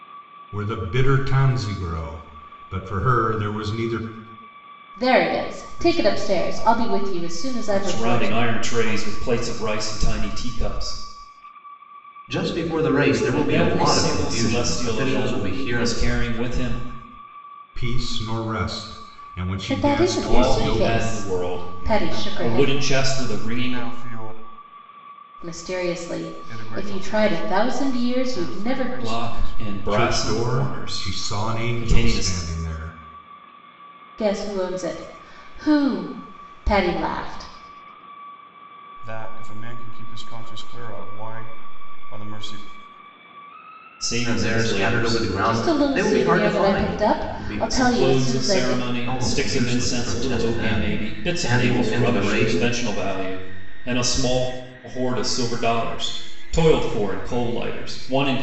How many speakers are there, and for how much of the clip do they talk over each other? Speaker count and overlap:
five, about 41%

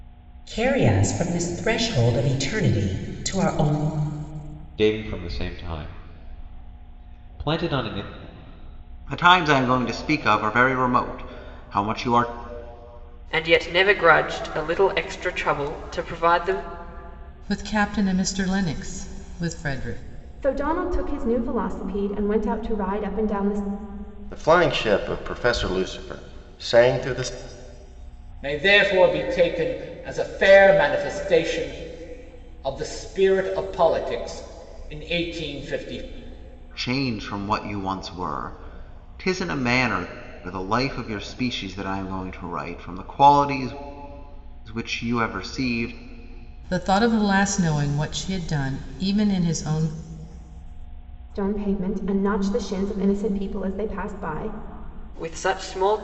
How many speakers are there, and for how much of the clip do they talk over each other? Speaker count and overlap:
eight, no overlap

